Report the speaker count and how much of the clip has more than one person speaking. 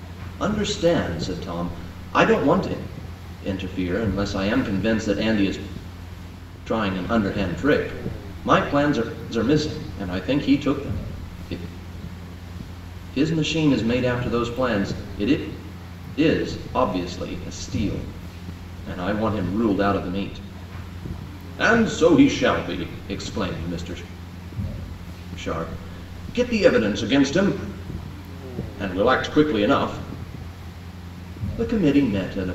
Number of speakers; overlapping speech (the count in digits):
1, no overlap